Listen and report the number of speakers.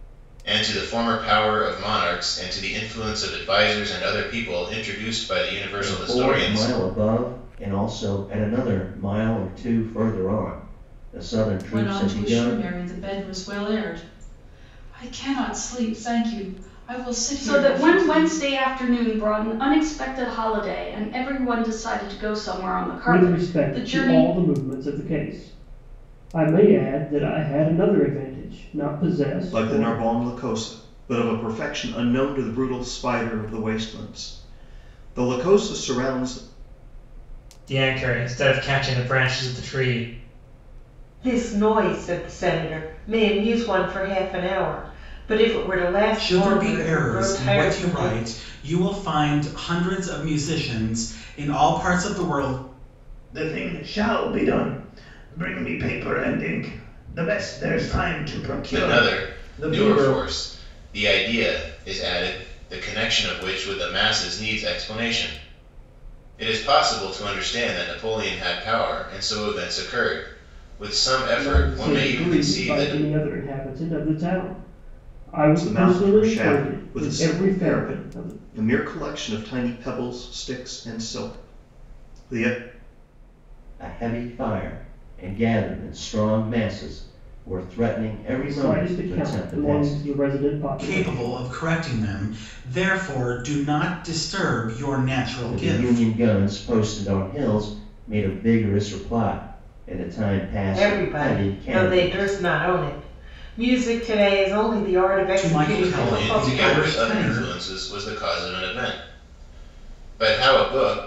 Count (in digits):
10